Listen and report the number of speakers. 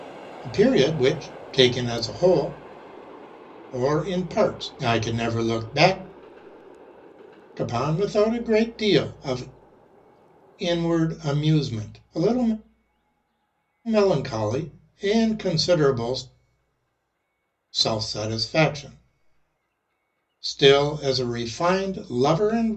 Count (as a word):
one